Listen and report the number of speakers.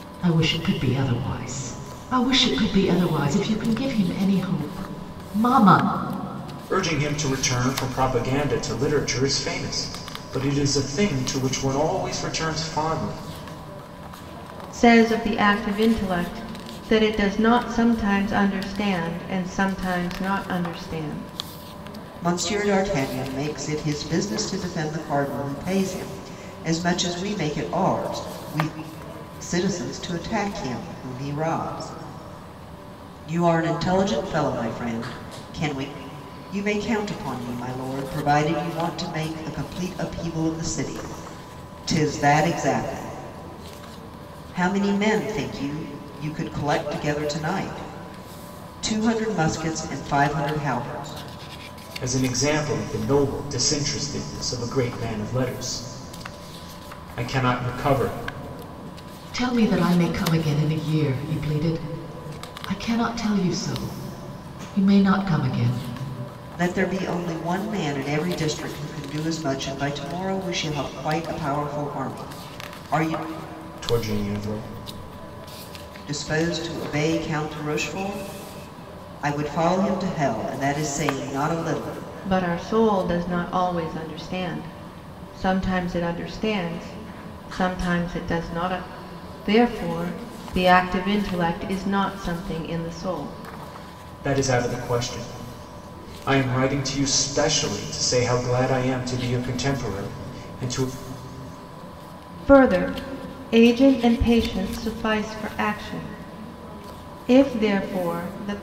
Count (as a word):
four